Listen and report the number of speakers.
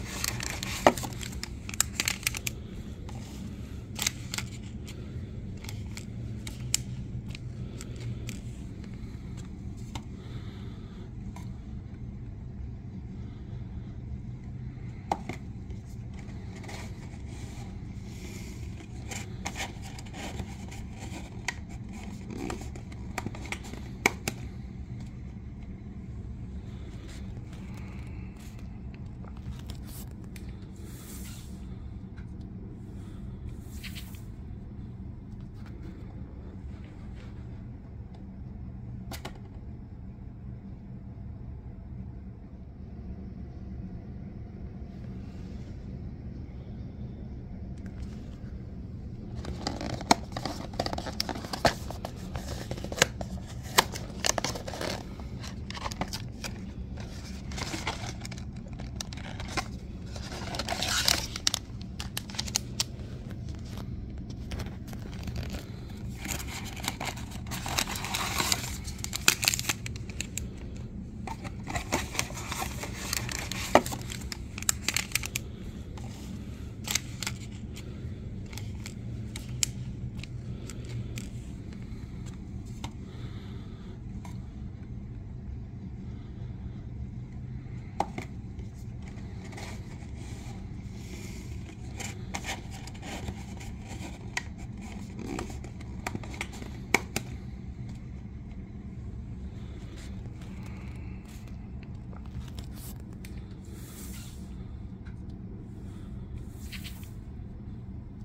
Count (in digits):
0